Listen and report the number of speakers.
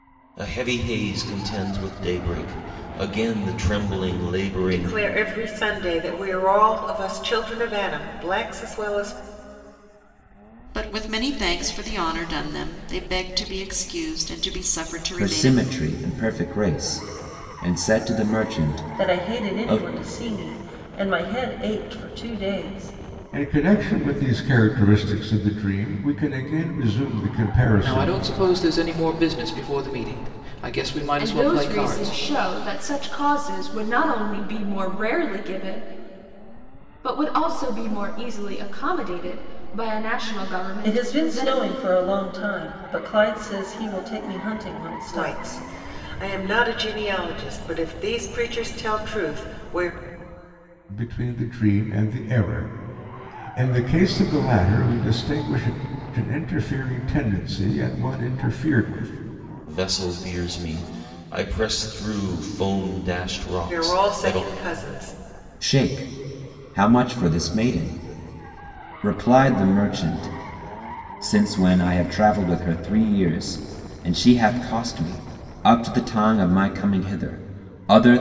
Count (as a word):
eight